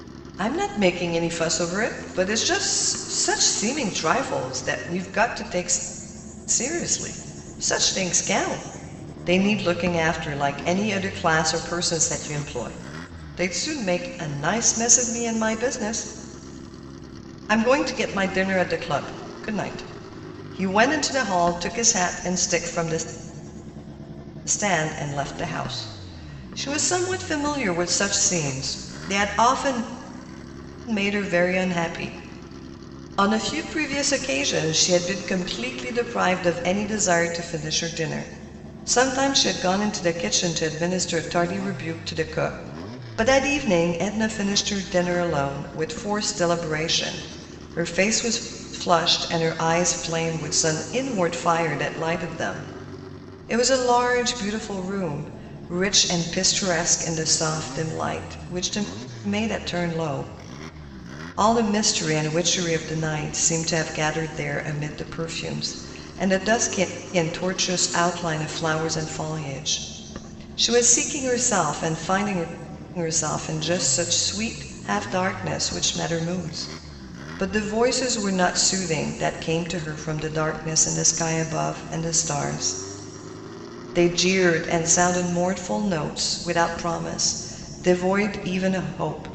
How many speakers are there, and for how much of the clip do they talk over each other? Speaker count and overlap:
1, no overlap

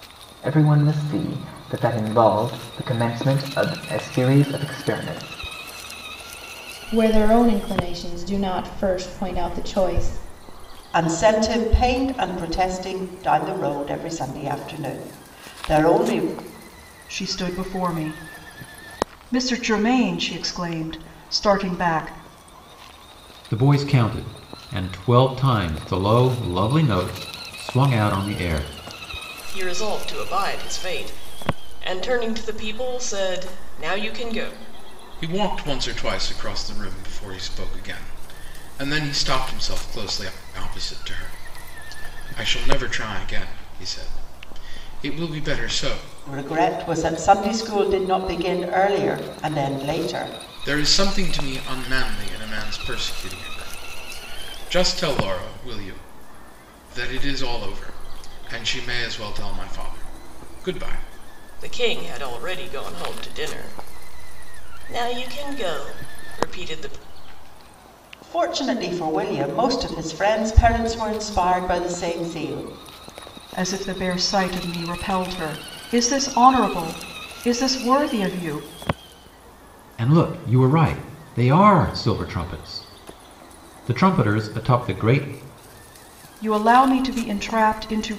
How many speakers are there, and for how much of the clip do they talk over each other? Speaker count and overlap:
7, no overlap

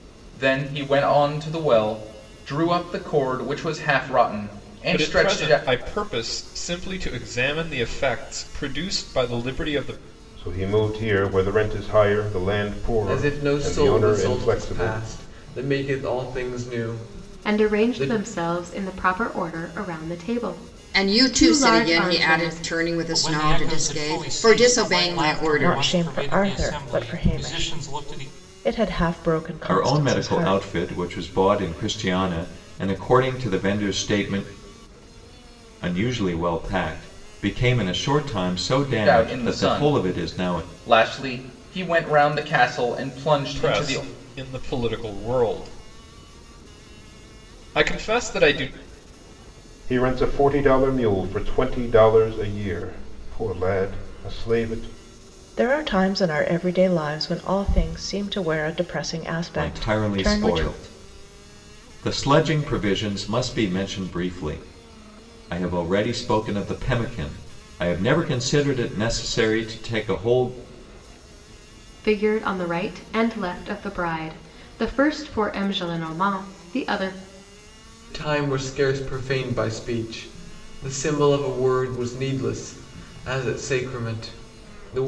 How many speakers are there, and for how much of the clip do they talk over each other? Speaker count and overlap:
9, about 18%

